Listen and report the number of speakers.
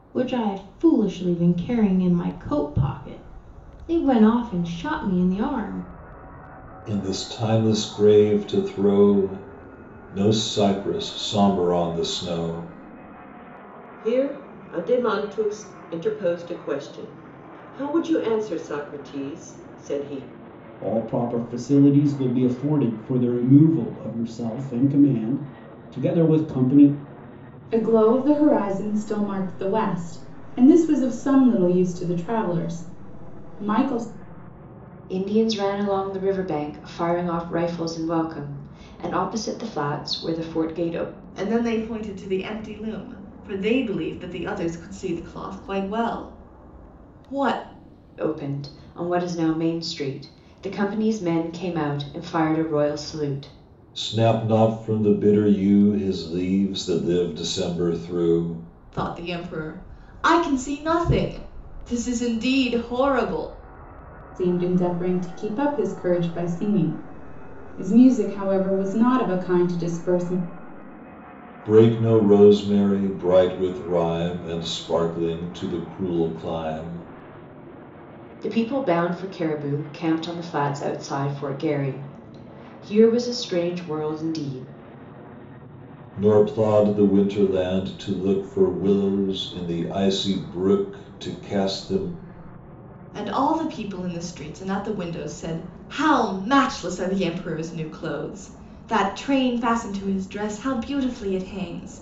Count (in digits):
7